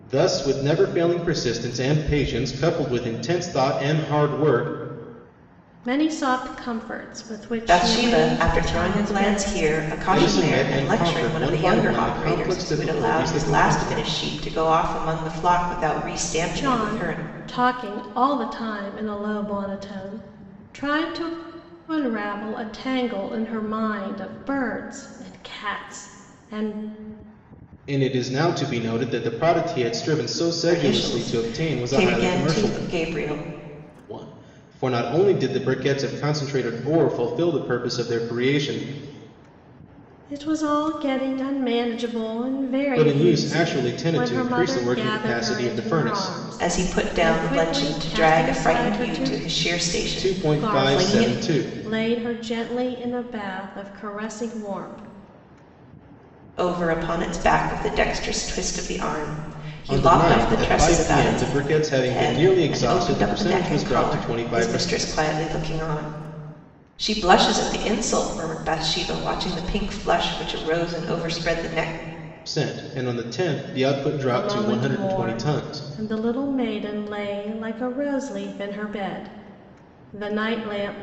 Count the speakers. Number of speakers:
3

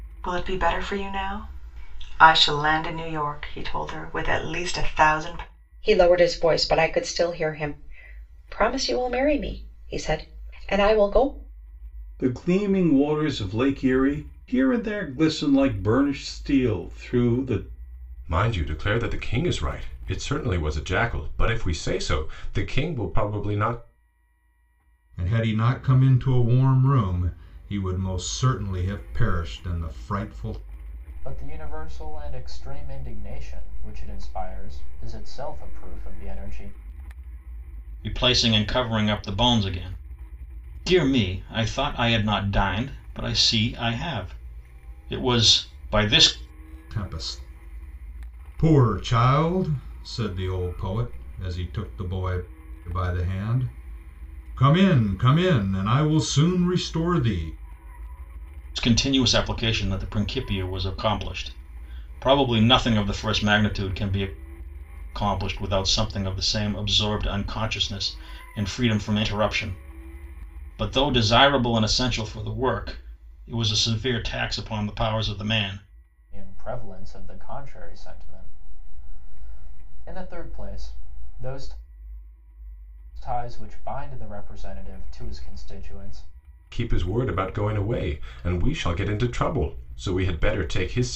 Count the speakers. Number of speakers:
7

